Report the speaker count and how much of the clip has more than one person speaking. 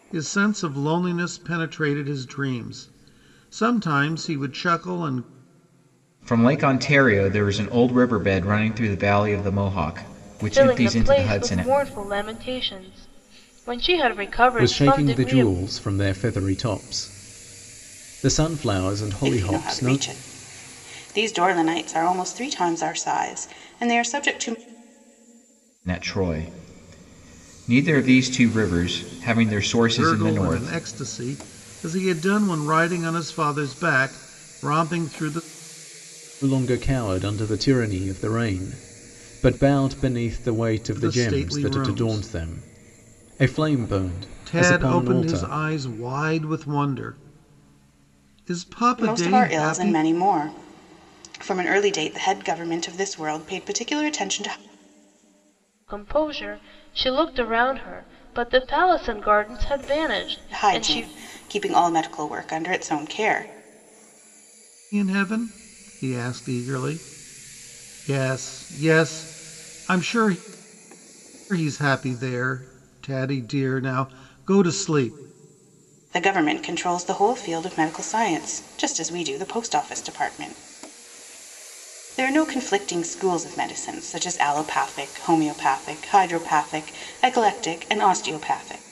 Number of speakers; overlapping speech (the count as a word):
five, about 9%